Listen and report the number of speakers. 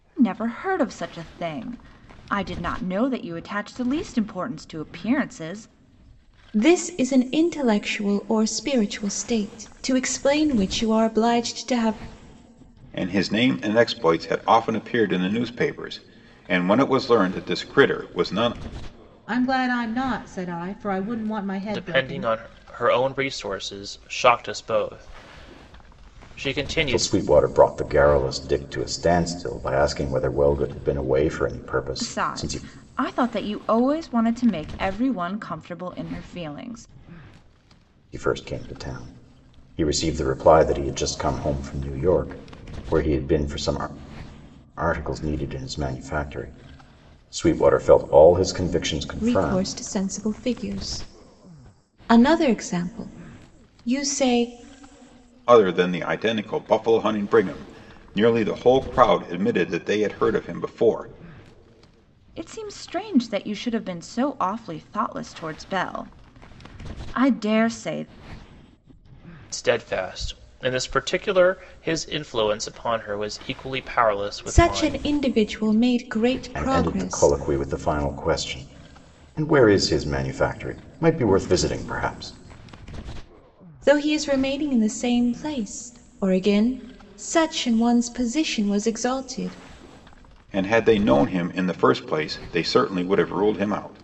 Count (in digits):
6